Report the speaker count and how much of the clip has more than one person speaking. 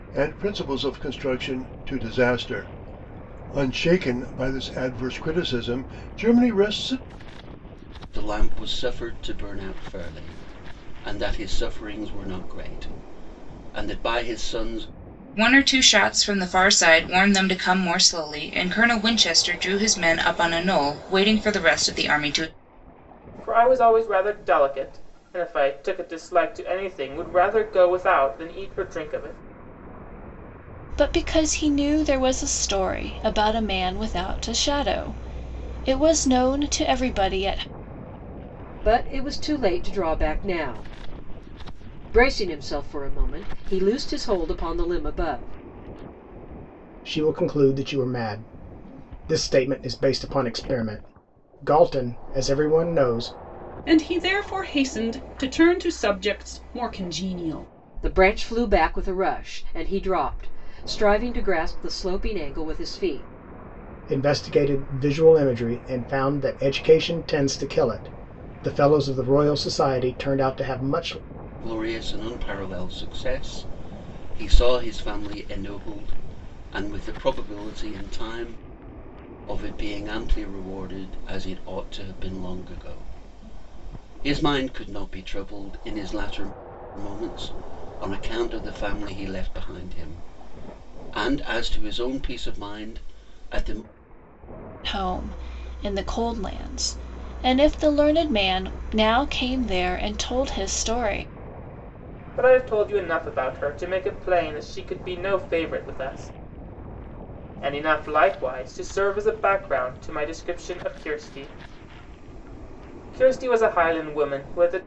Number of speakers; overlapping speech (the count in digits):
8, no overlap